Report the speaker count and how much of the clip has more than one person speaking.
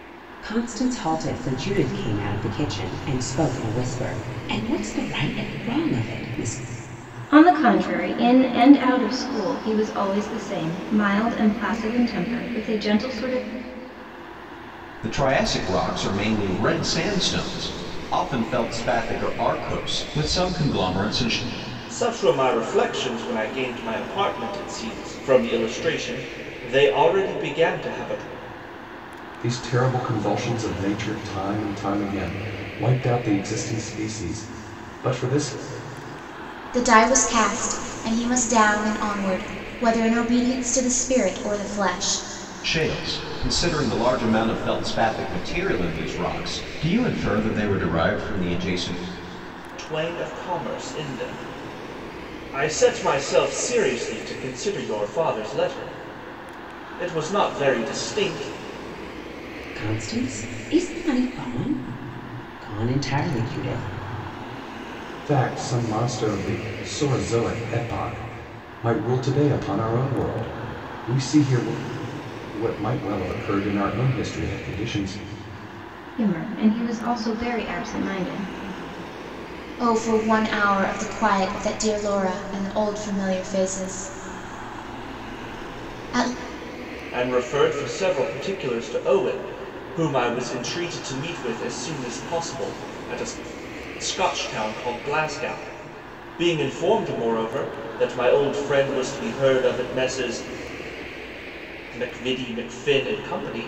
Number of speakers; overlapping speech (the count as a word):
six, no overlap